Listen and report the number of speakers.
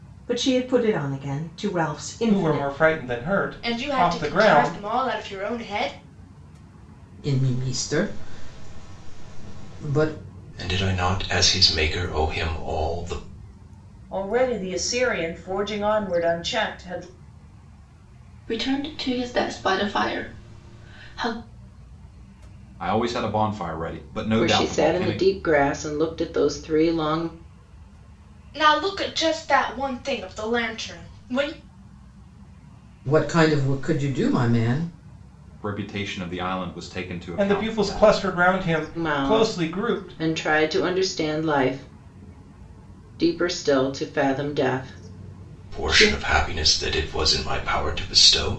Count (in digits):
9